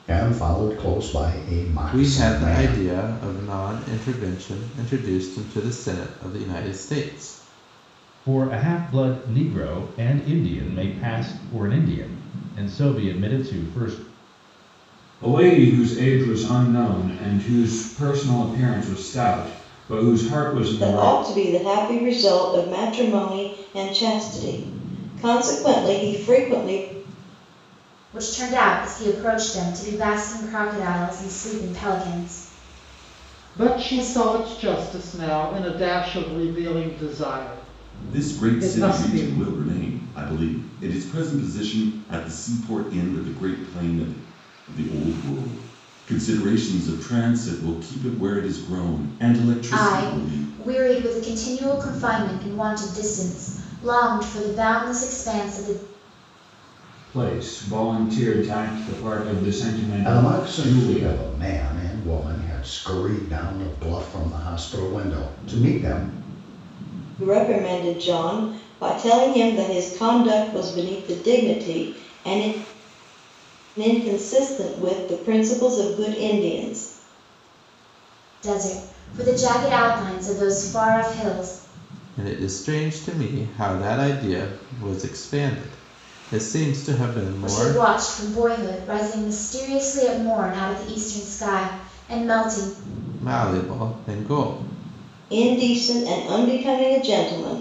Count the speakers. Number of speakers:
8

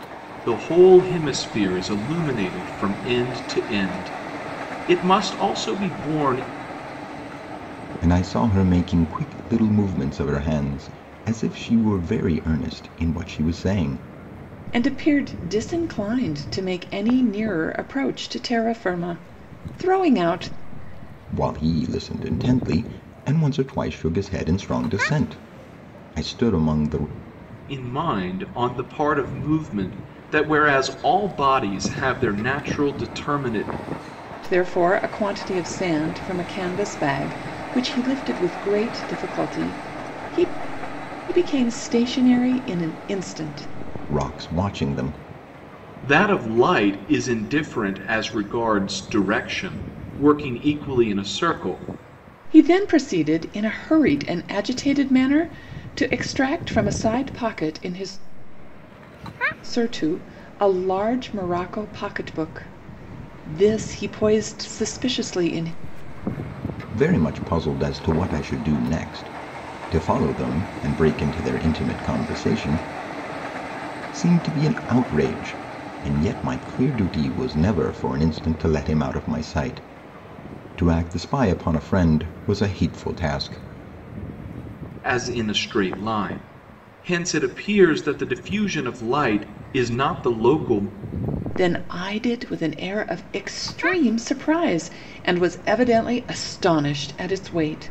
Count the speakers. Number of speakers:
3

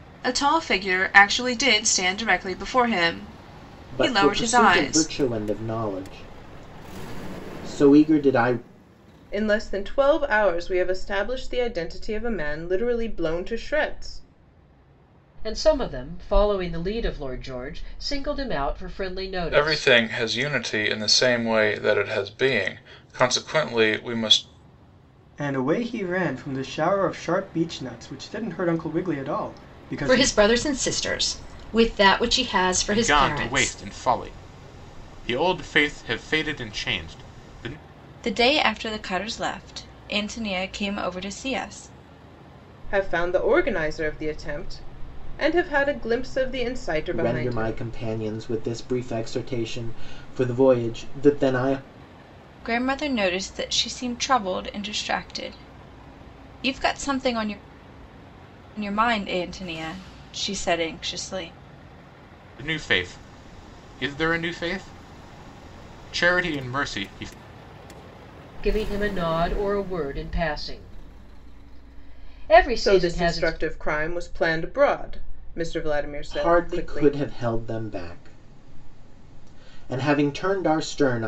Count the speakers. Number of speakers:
9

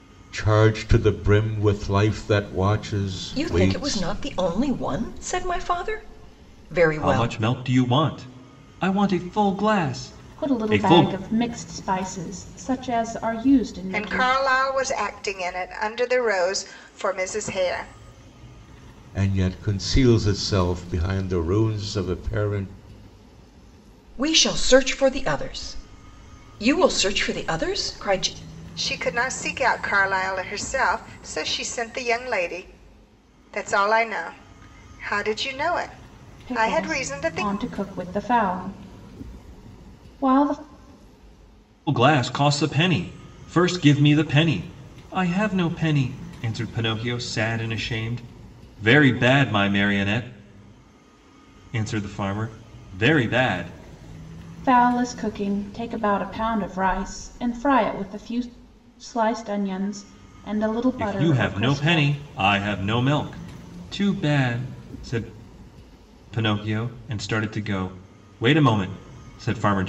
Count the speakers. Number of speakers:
5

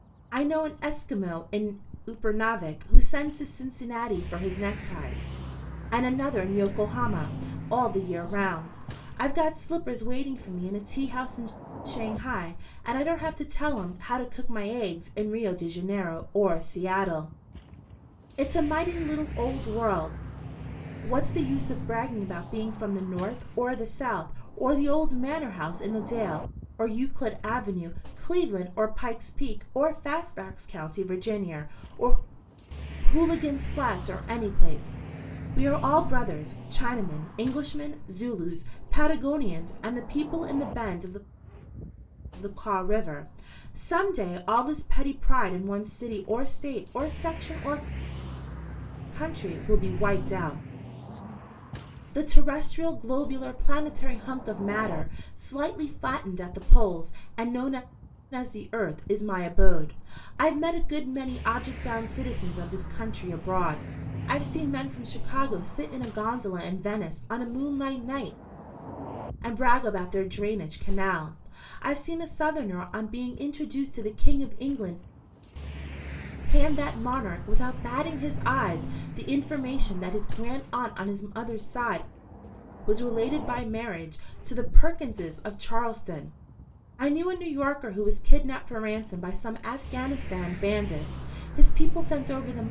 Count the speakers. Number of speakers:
1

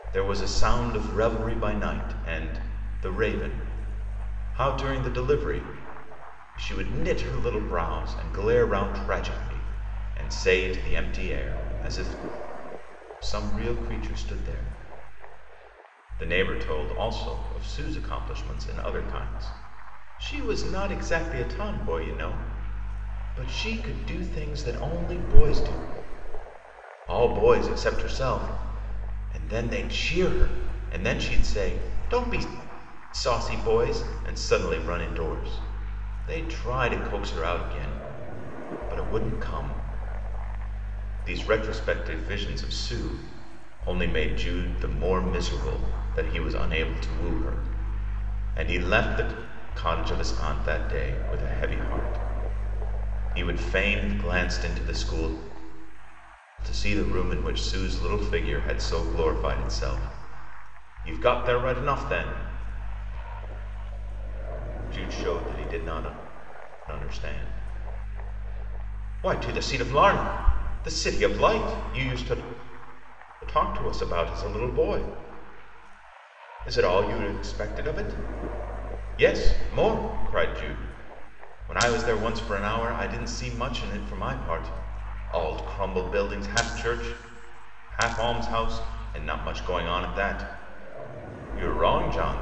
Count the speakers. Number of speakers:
1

